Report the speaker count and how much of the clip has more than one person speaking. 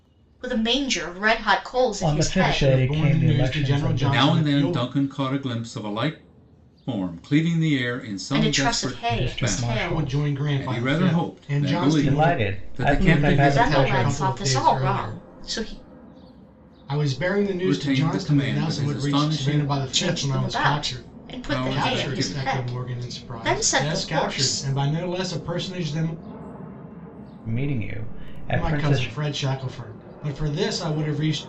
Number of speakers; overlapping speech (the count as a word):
four, about 54%